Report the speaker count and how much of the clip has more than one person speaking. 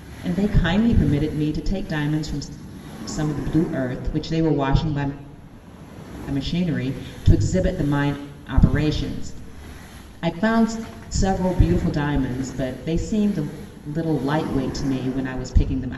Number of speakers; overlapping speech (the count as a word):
one, no overlap